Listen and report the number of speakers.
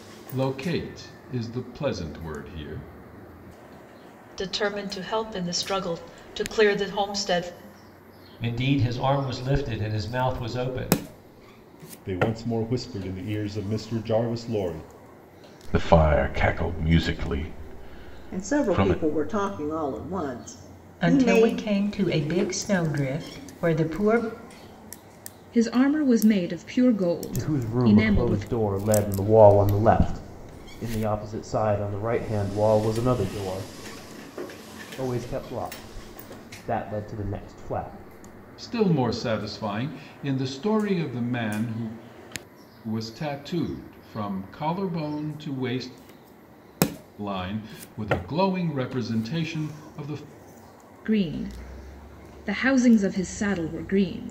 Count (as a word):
nine